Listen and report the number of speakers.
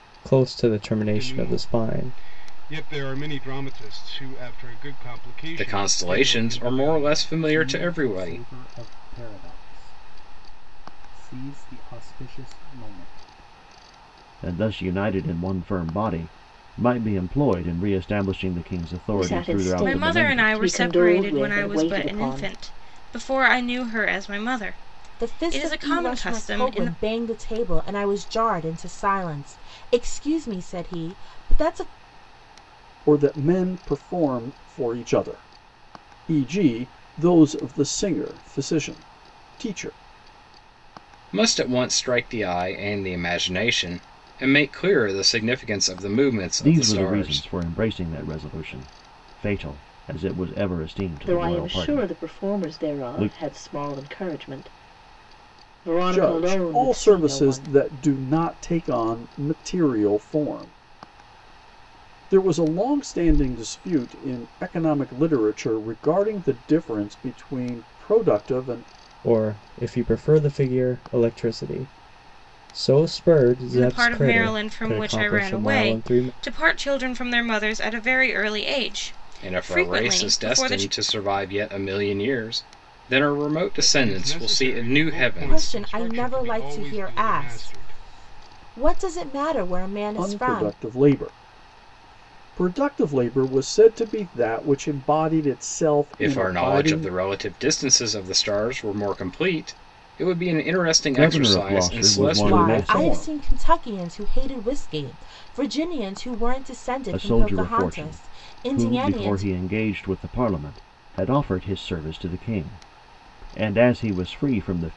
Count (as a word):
nine